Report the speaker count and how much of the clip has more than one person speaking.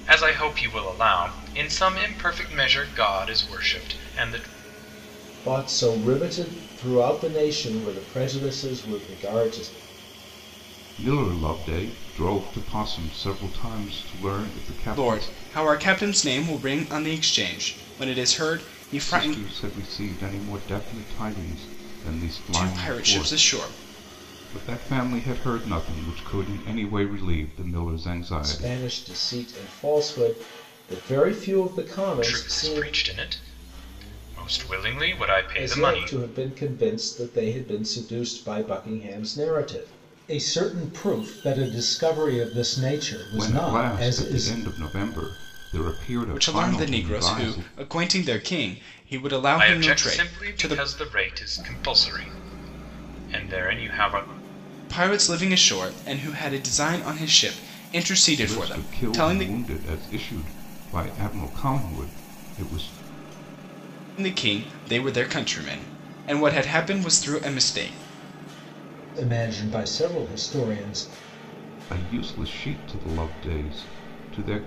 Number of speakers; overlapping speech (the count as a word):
four, about 12%